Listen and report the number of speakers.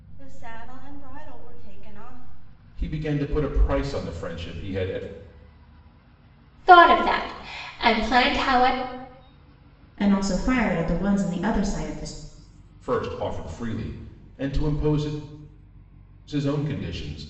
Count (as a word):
four